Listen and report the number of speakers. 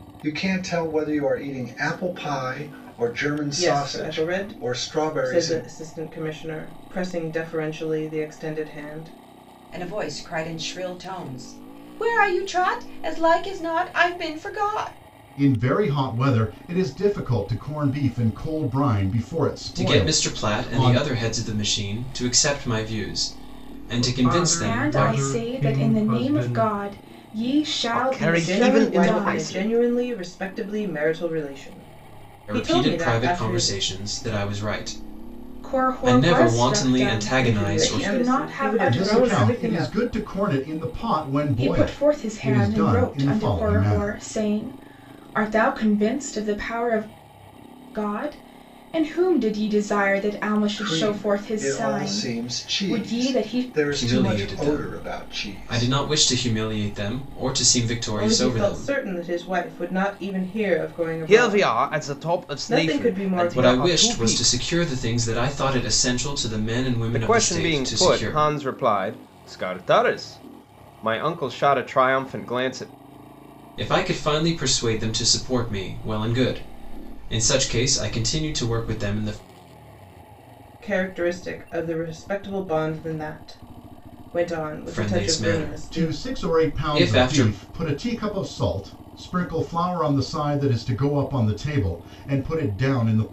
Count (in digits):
8